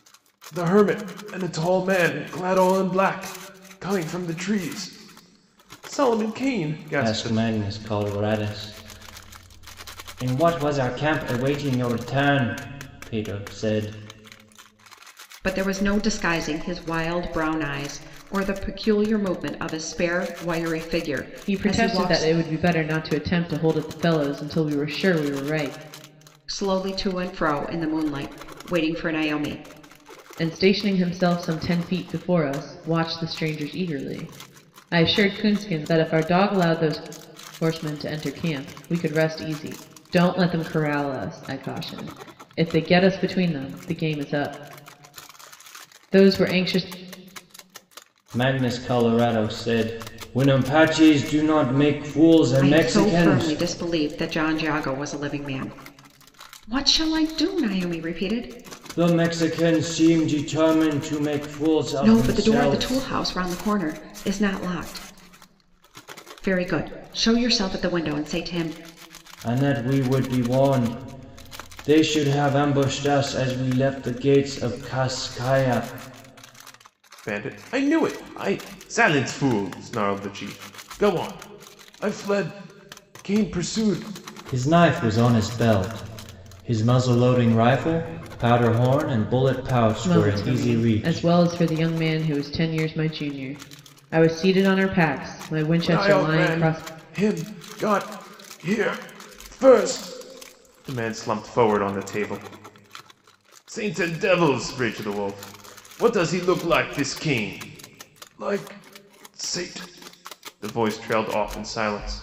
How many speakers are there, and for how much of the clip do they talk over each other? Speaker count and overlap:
4, about 5%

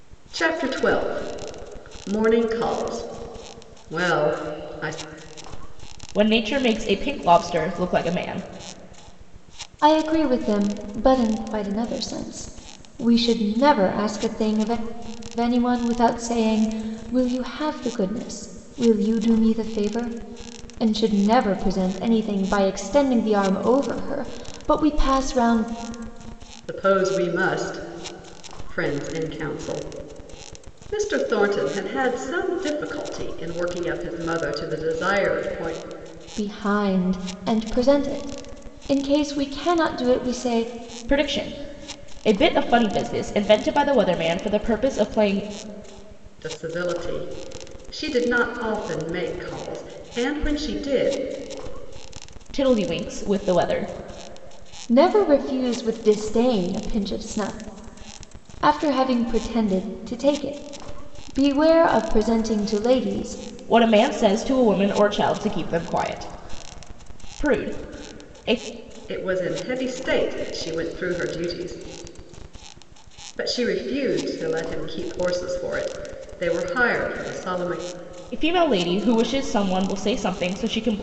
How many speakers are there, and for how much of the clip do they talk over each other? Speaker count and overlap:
3, no overlap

